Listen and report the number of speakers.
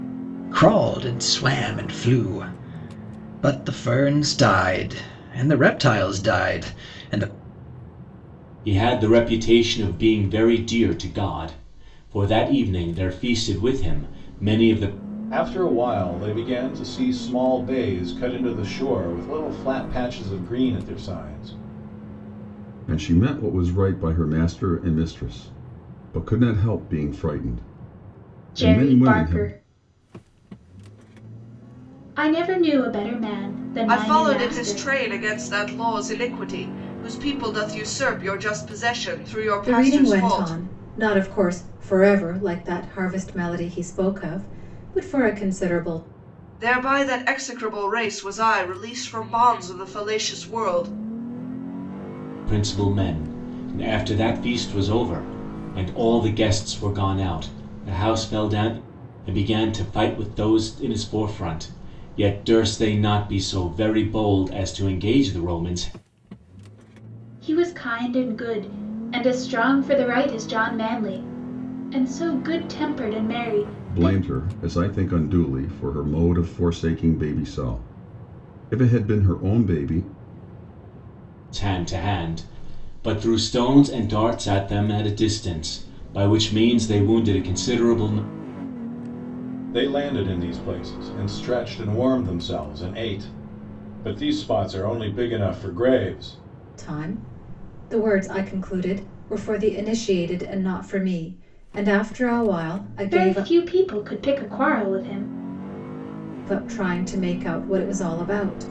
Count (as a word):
seven